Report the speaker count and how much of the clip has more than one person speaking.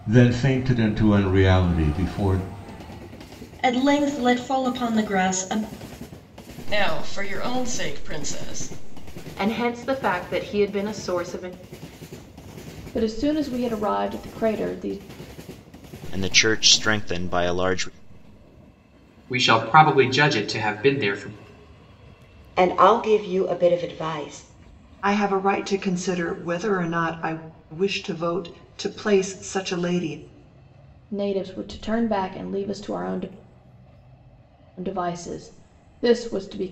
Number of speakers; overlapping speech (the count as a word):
nine, no overlap